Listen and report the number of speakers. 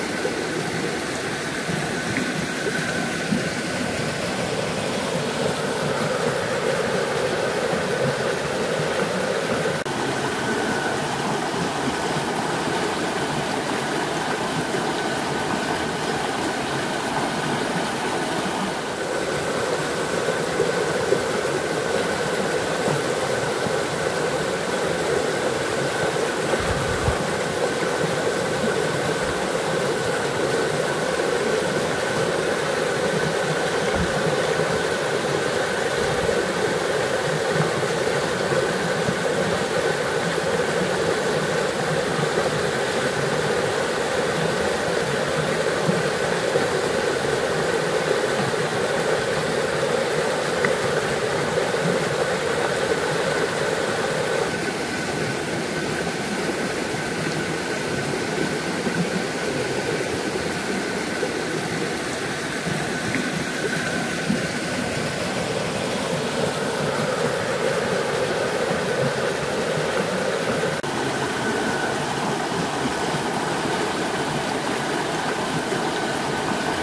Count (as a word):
zero